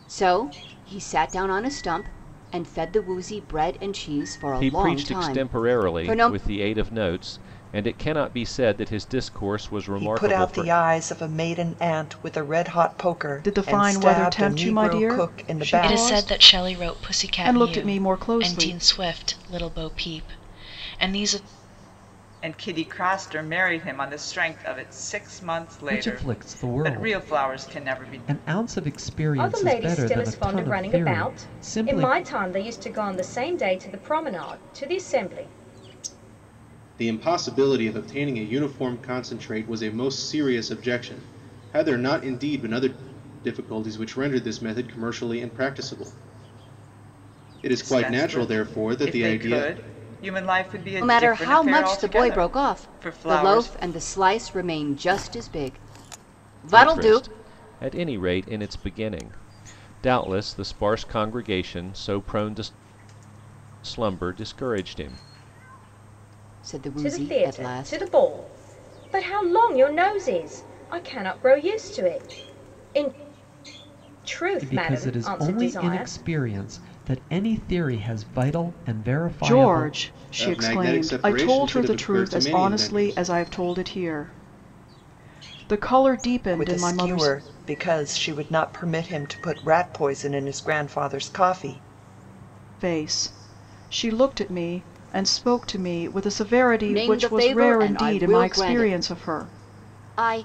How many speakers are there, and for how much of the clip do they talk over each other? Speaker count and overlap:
nine, about 28%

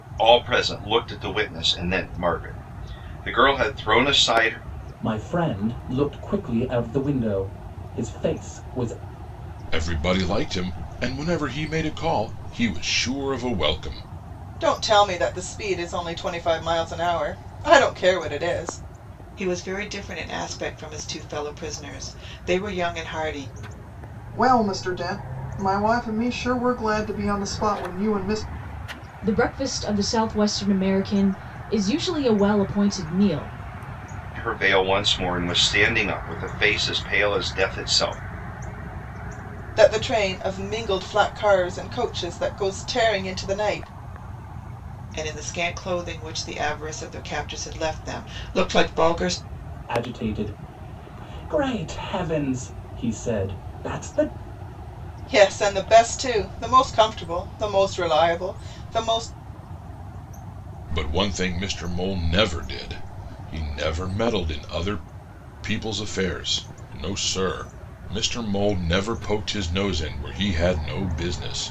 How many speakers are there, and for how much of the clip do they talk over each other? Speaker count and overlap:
seven, no overlap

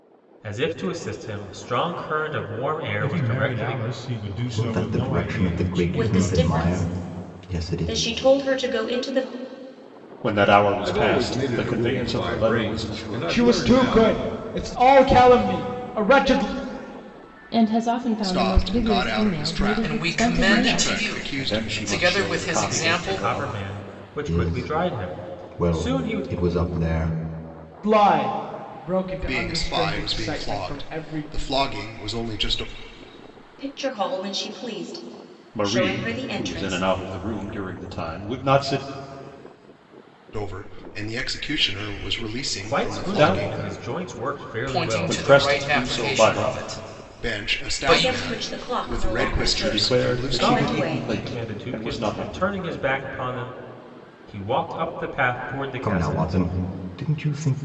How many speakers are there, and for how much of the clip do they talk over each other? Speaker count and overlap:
ten, about 50%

